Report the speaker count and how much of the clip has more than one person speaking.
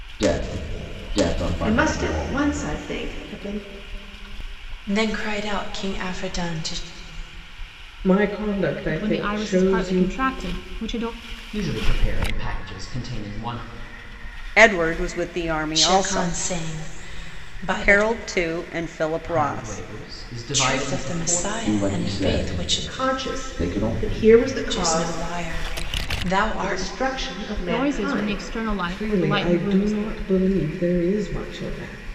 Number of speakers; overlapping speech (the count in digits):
7, about 30%